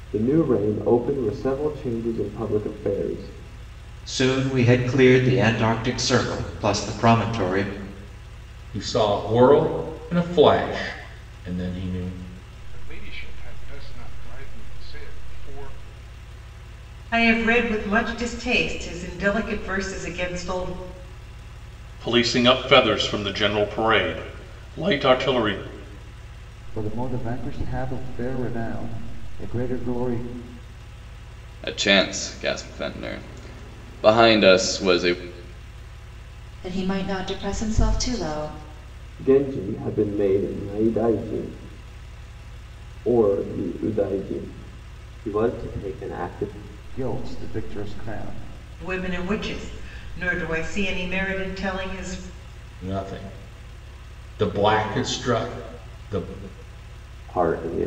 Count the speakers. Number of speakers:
nine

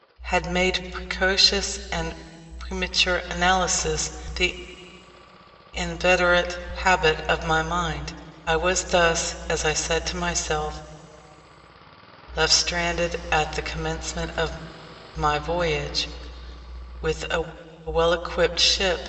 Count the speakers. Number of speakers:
one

